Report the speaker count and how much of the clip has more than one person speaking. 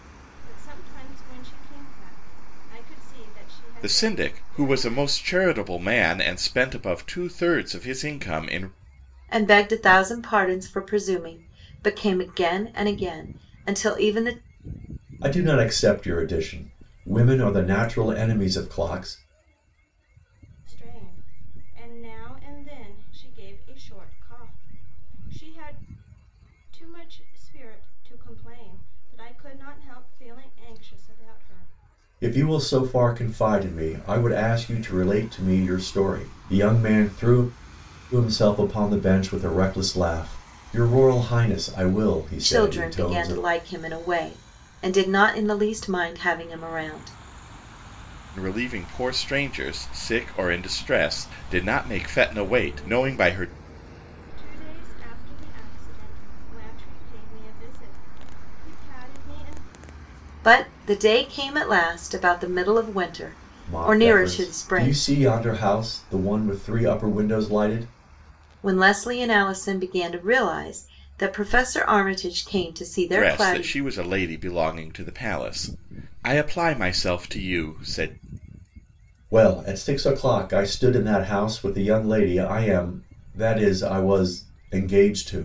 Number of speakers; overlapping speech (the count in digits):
4, about 5%